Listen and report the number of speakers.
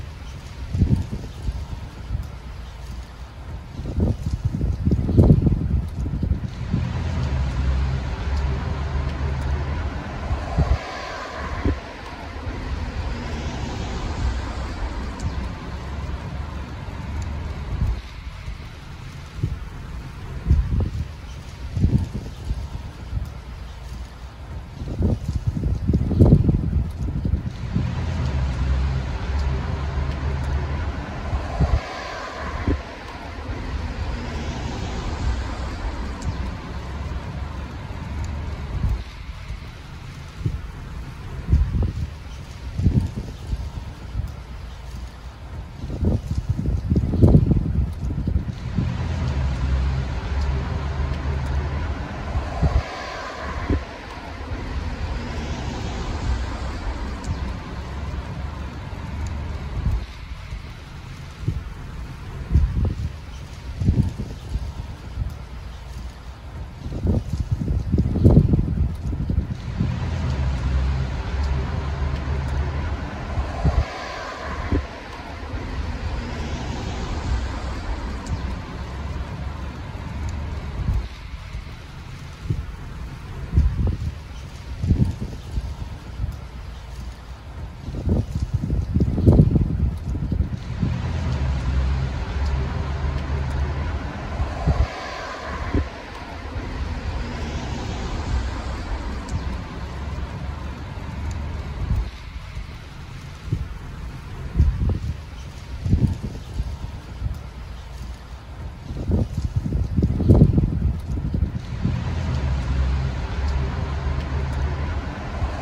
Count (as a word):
zero